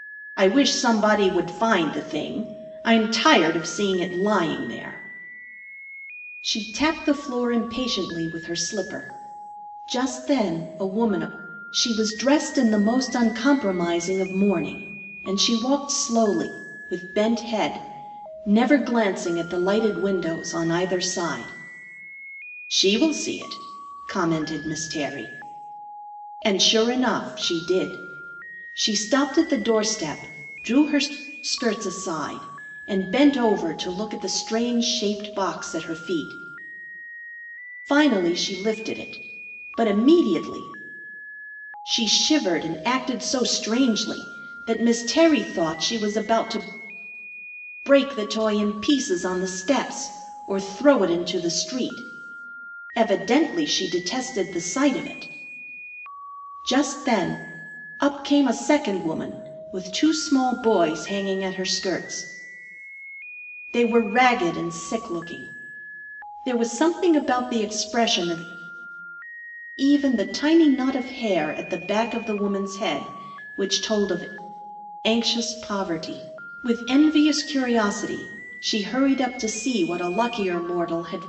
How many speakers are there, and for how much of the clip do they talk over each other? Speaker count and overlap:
1, no overlap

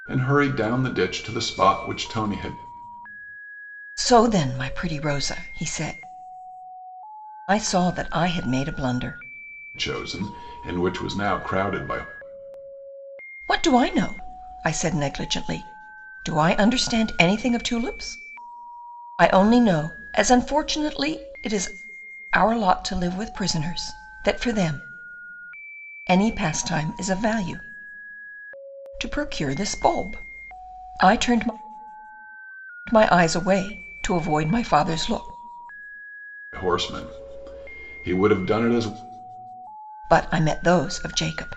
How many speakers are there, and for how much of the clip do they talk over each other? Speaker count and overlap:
2, no overlap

